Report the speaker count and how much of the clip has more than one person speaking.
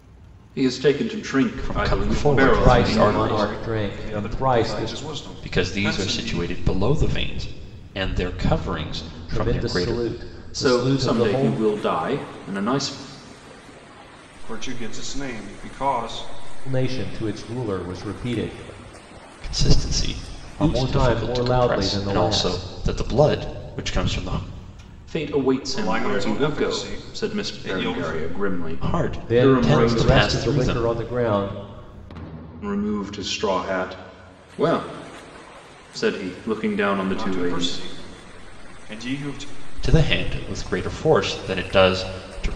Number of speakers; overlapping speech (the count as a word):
four, about 33%